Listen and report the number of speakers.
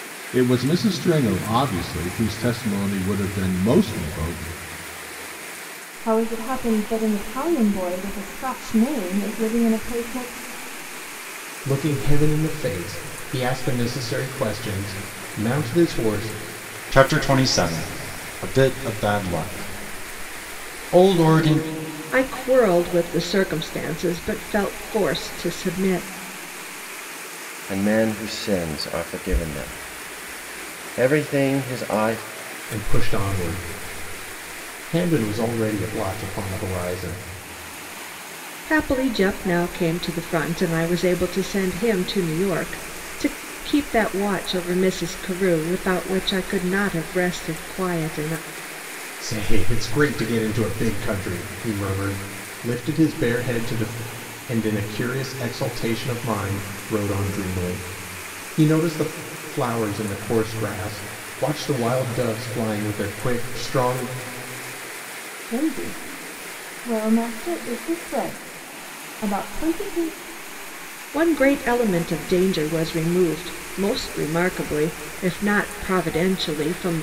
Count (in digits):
6